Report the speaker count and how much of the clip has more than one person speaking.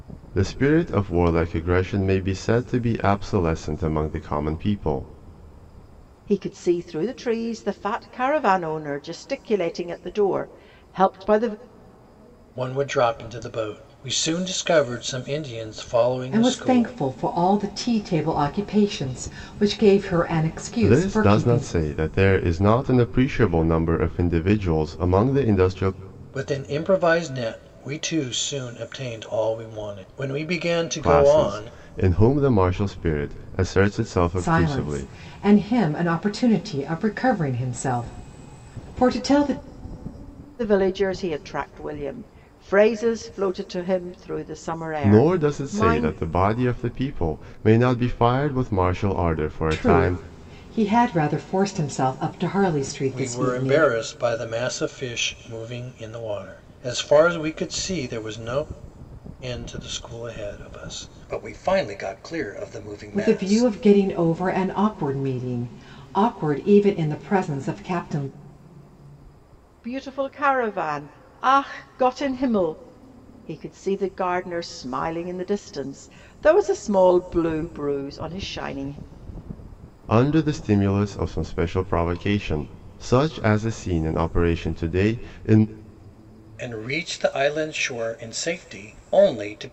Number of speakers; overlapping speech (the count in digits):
4, about 7%